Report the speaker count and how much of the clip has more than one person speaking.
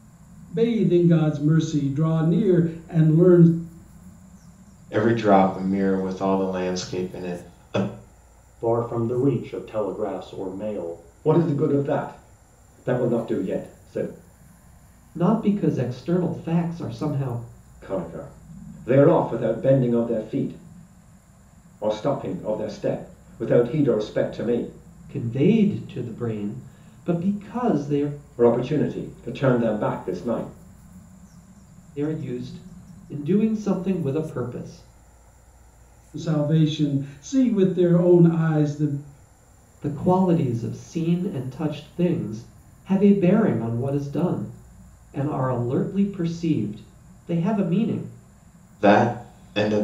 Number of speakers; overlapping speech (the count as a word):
five, no overlap